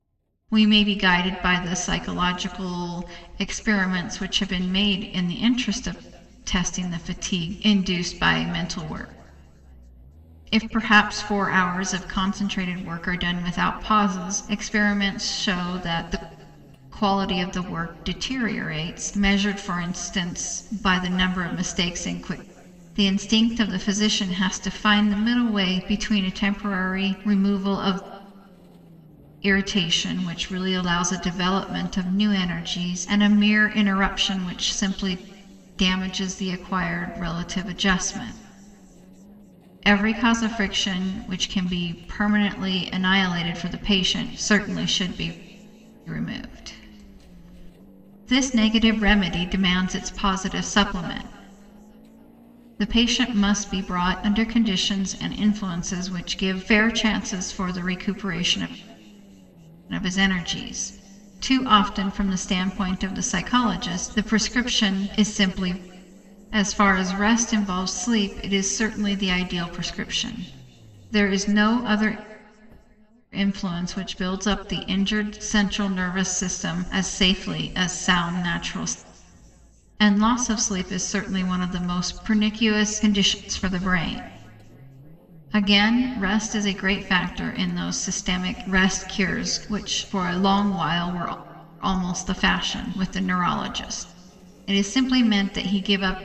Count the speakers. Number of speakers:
one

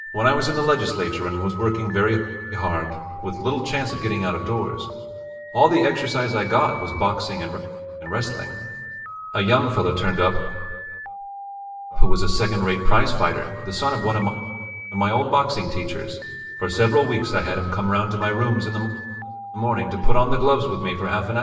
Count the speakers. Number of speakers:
one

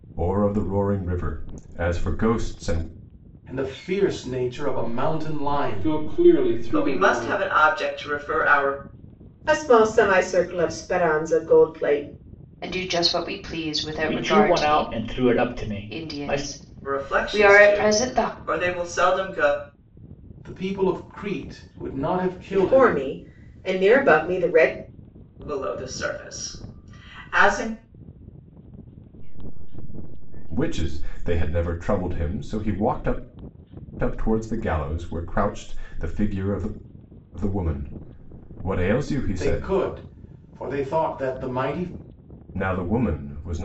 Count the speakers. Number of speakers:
eight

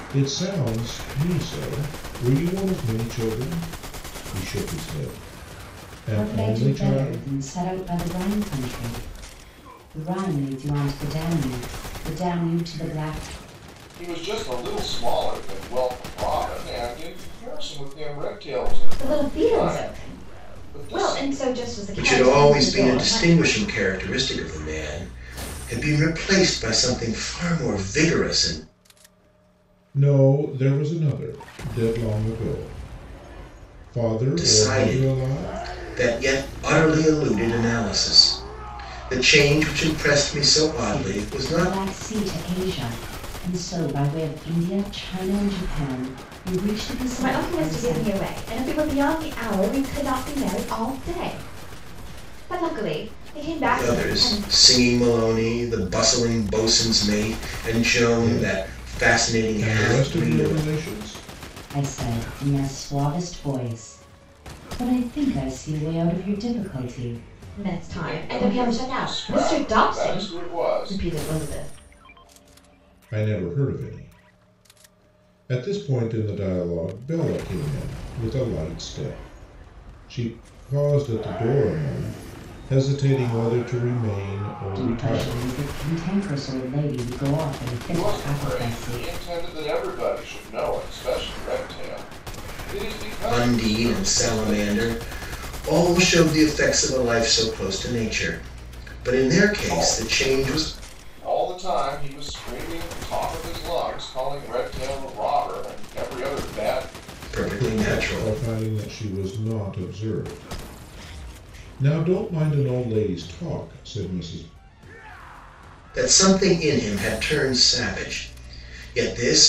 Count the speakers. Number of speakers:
five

